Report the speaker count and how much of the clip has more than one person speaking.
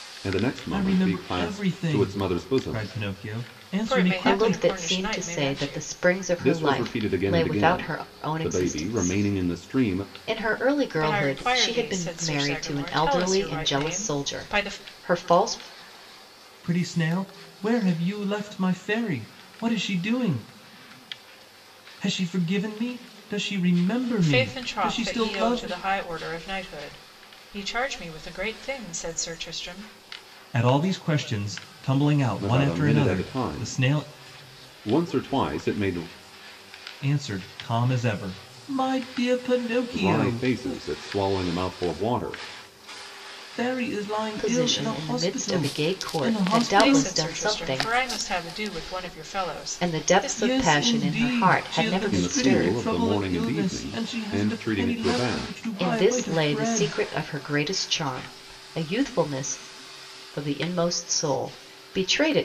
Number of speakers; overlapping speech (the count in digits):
4, about 42%